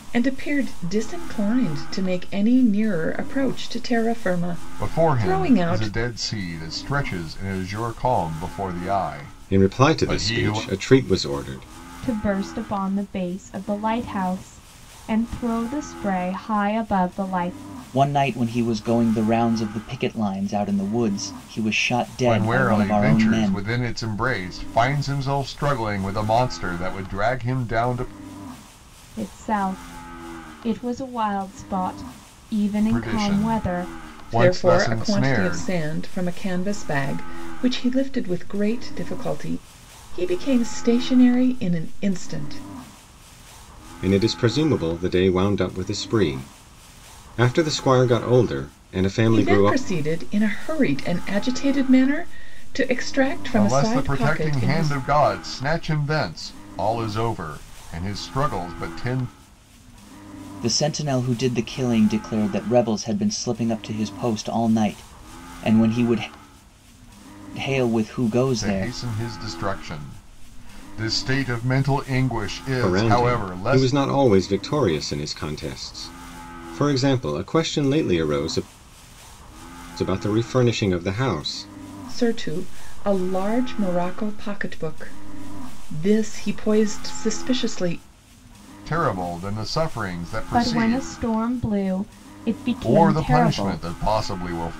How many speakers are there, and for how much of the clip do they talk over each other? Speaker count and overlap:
5, about 12%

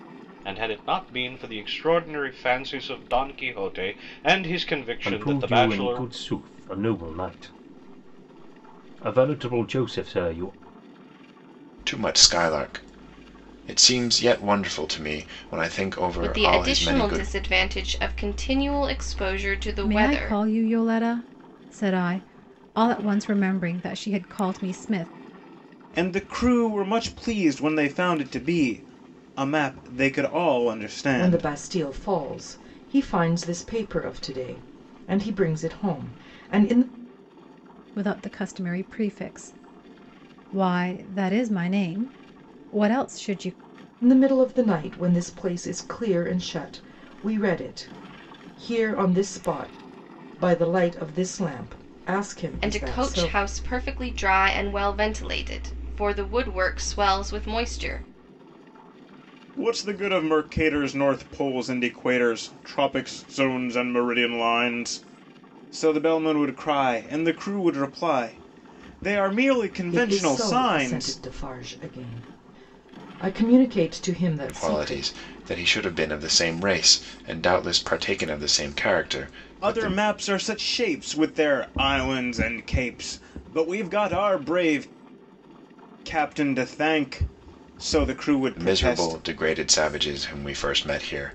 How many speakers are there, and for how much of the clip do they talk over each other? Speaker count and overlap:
7, about 8%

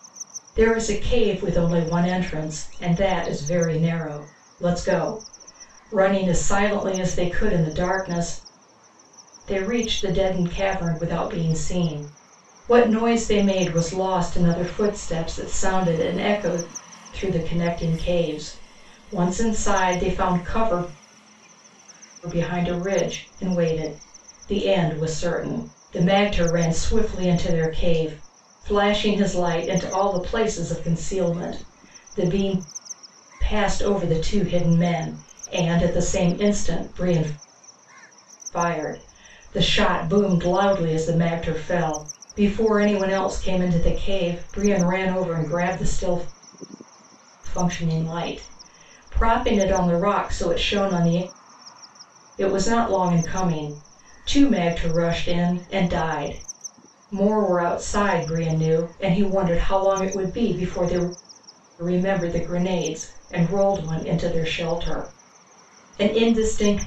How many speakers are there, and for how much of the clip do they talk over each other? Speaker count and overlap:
1, no overlap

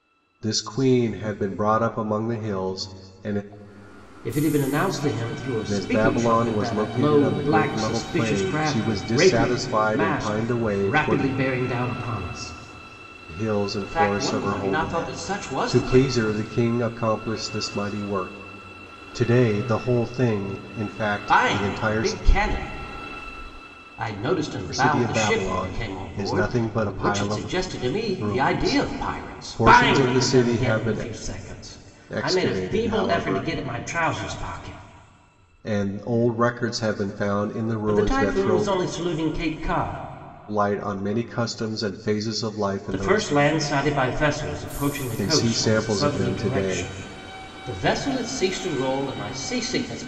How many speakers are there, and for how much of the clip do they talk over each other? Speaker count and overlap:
2, about 38%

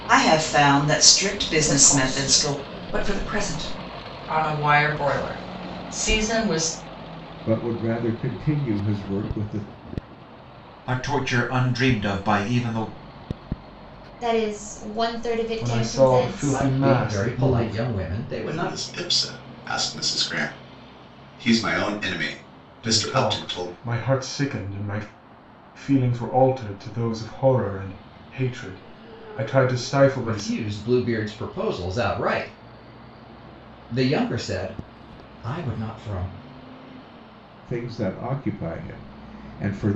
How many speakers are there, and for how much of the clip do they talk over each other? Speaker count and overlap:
9, about 13%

